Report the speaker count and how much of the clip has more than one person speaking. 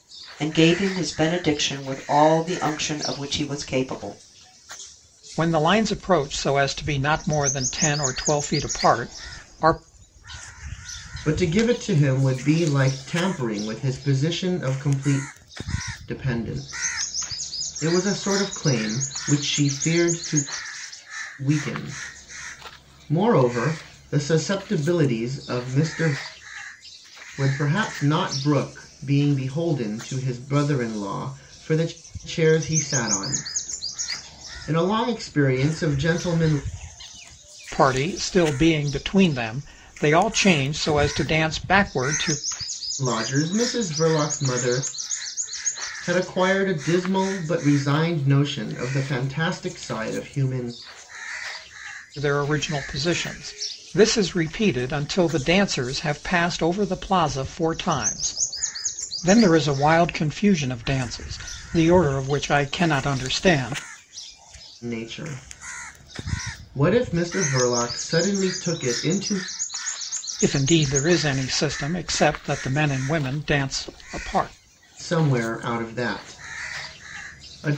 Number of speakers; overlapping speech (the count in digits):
3, no overlap